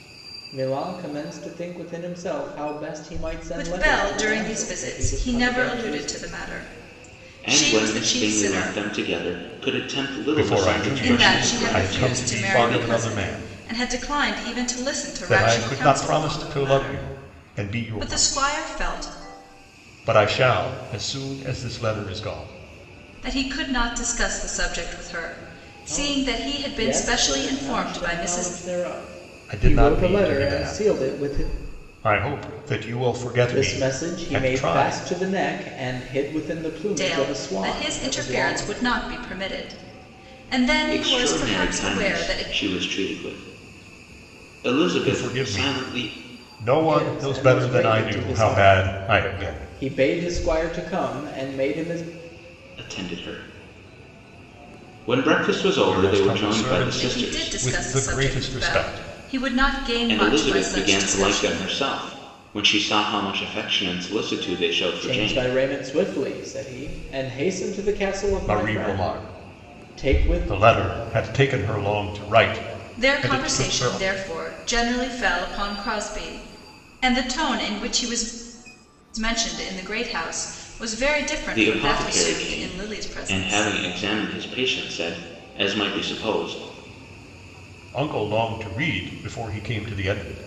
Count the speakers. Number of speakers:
four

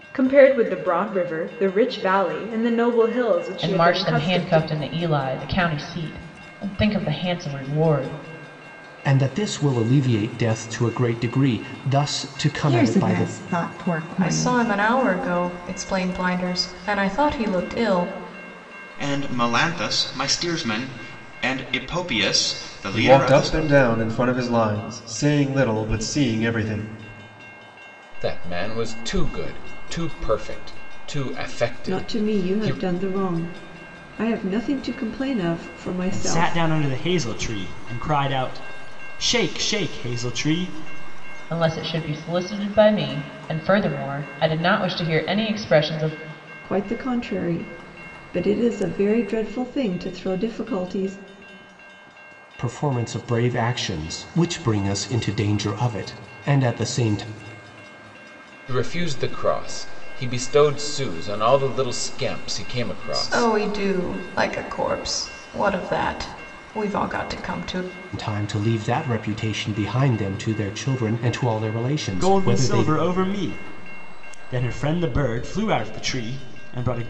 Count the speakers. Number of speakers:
ten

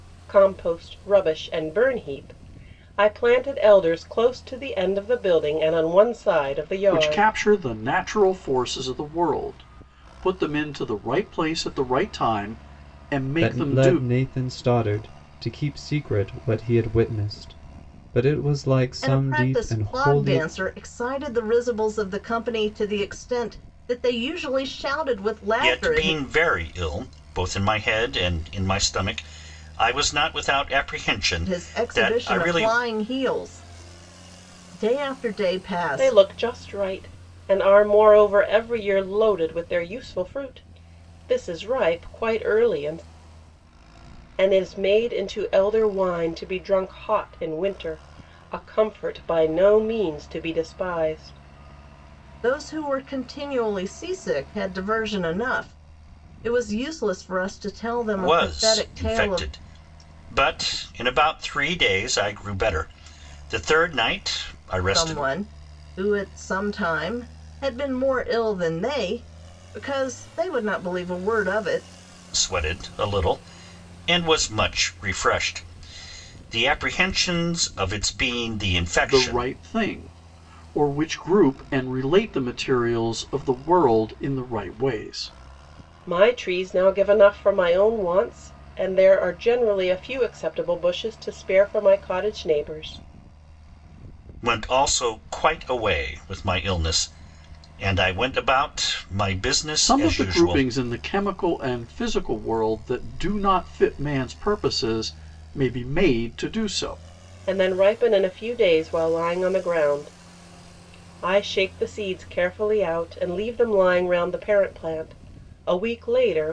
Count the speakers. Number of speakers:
five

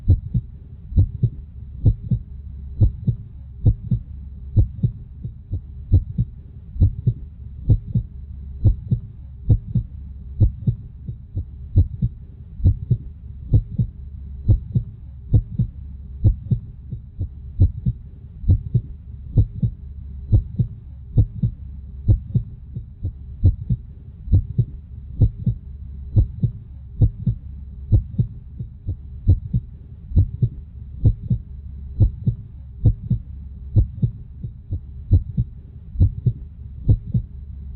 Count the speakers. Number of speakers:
zero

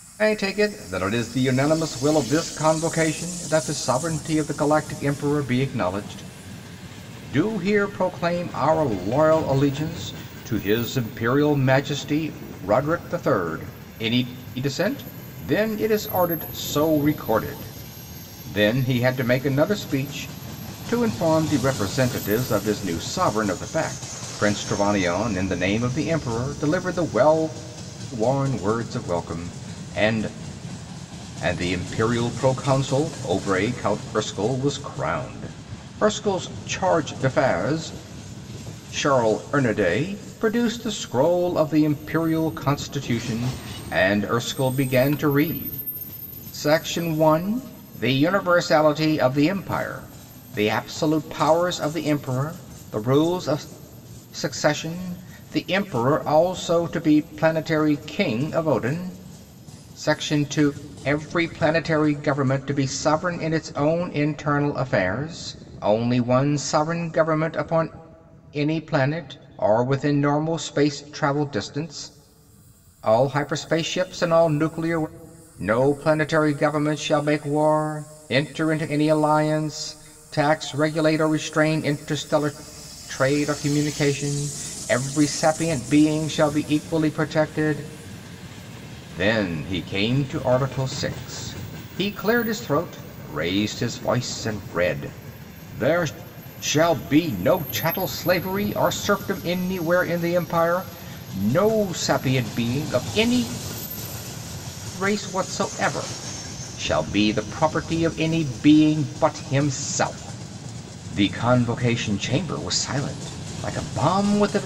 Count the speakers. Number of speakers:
one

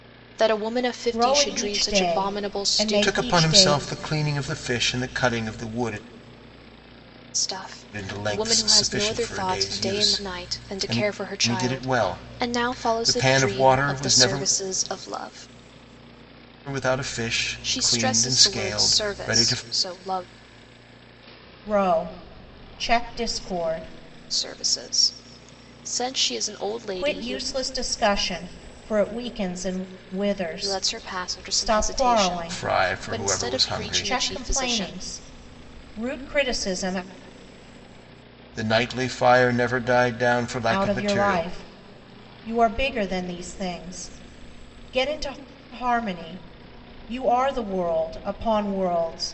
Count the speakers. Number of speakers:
three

